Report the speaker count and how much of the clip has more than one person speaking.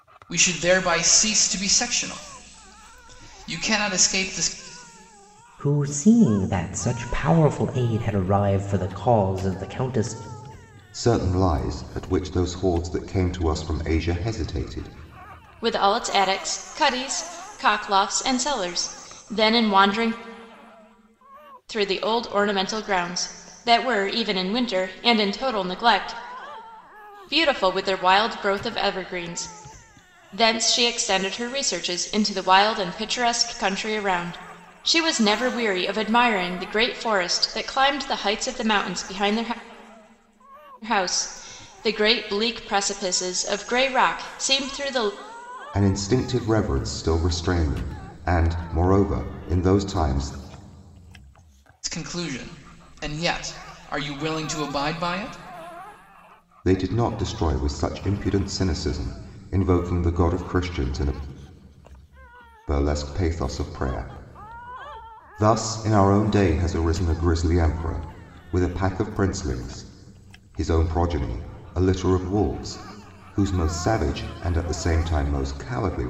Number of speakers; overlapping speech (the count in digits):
4, no overlap